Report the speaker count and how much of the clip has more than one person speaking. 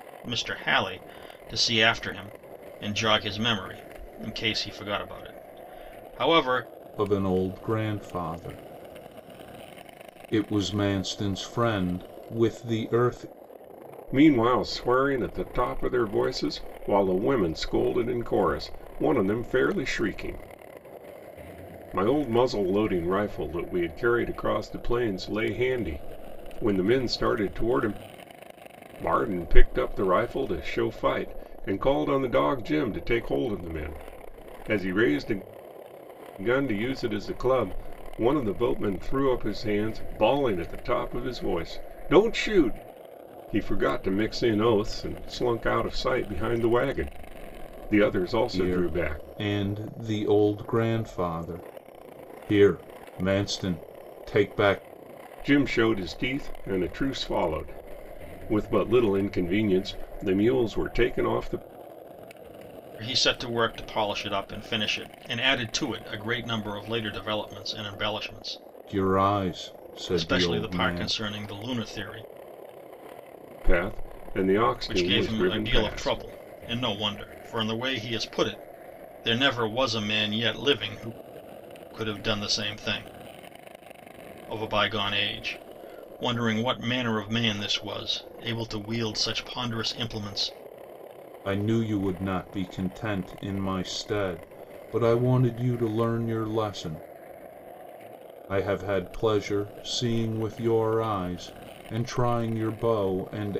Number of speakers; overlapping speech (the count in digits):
3, about 3%